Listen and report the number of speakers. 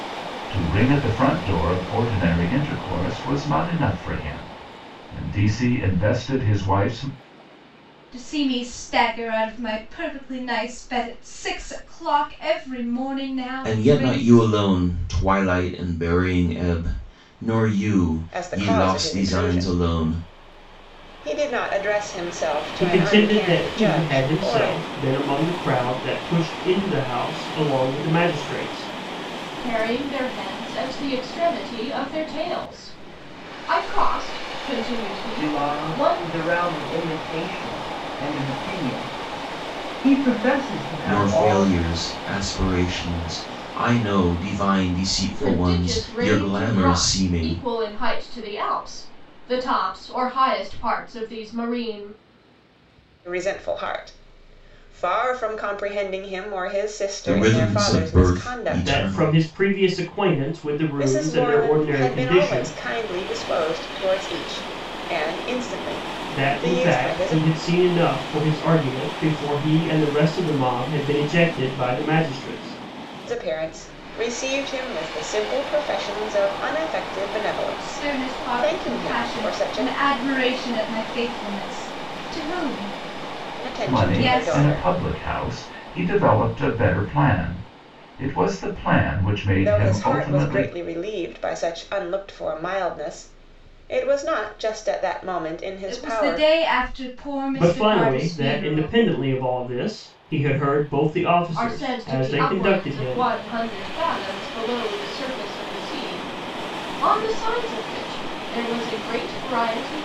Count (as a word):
seven